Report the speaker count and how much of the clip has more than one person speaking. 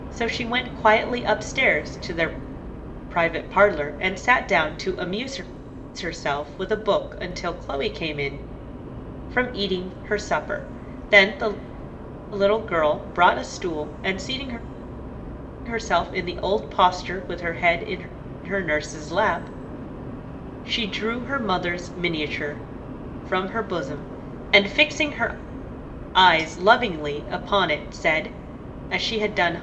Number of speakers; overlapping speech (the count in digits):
1, no overlap